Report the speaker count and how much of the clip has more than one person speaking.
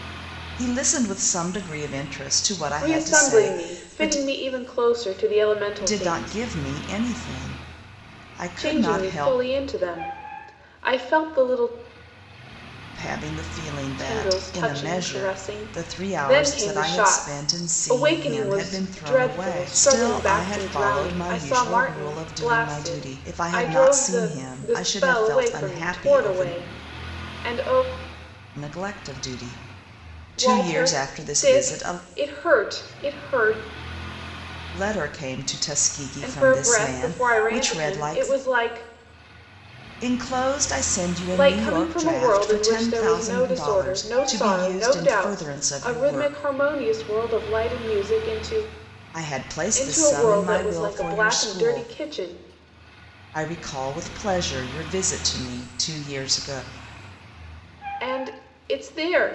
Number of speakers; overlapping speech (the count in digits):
2, about 44%